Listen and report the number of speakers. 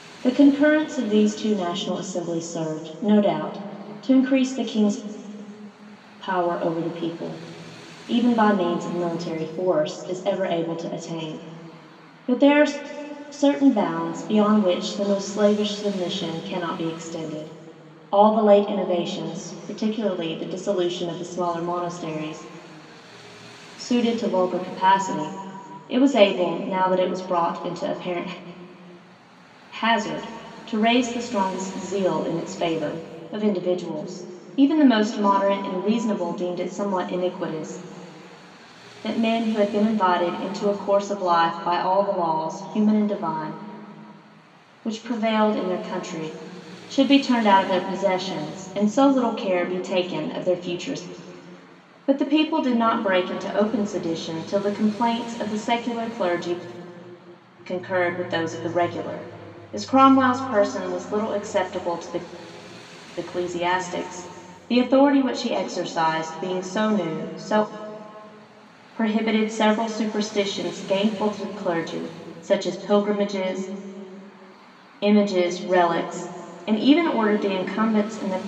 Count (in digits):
1